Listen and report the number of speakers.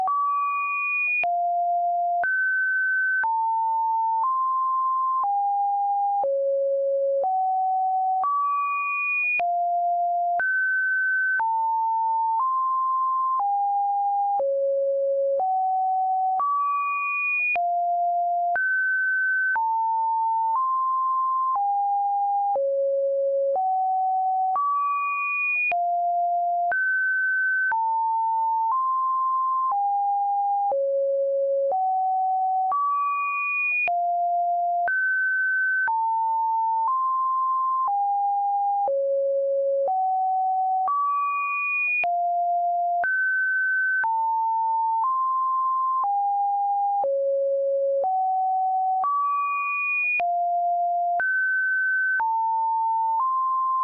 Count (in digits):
0